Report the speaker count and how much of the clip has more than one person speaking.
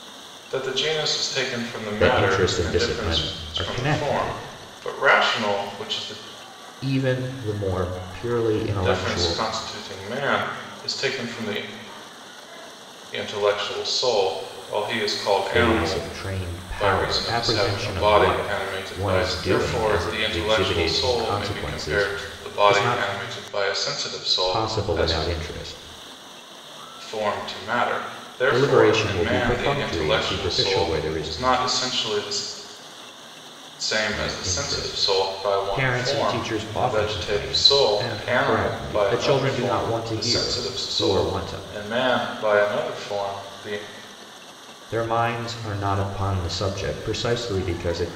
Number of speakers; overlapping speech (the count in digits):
2, about 44%